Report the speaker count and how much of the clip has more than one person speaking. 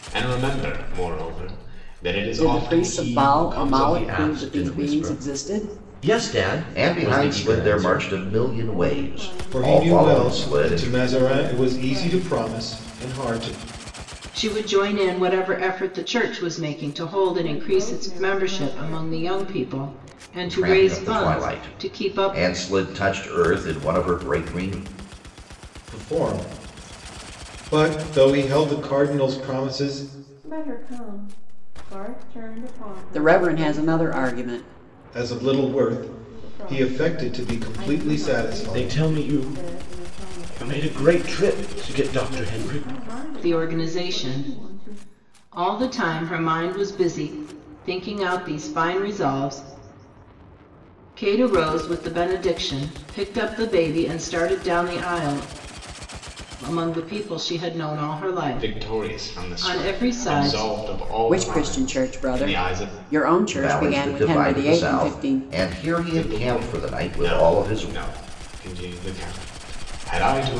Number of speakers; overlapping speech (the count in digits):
7, about 43%